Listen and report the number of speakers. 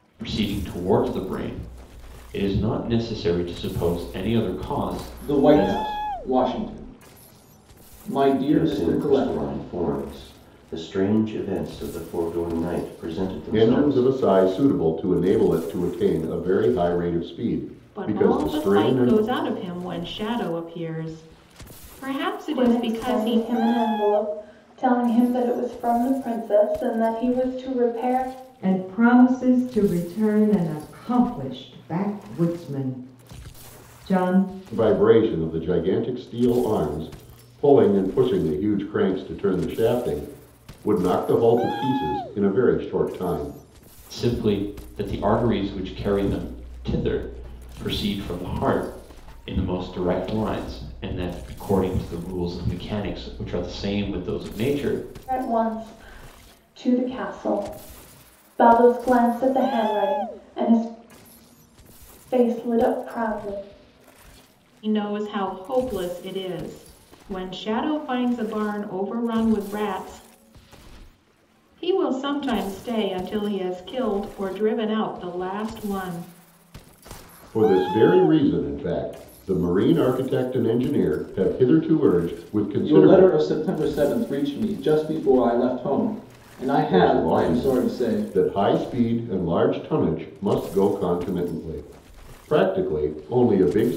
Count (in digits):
7